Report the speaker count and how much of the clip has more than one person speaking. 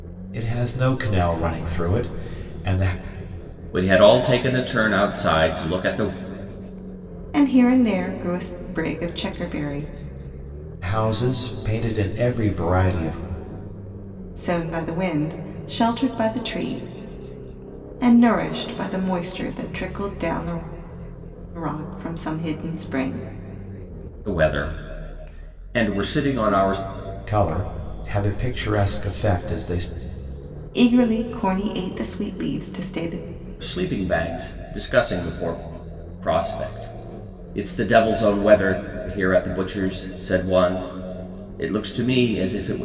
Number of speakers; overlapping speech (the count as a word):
three, no overlap